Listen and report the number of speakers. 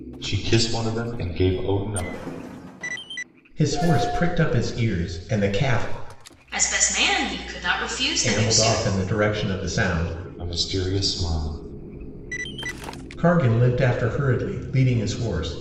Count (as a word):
three